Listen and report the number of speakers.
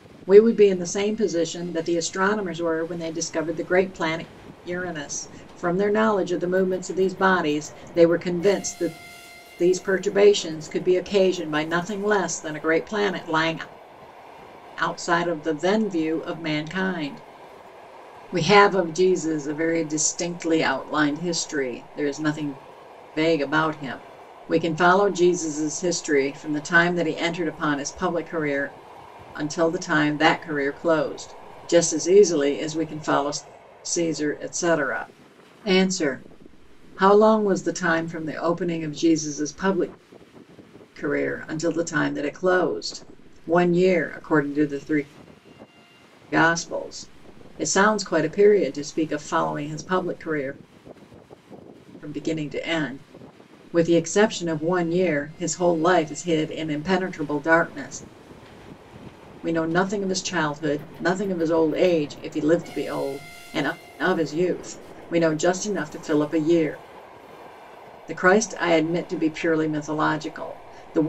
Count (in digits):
1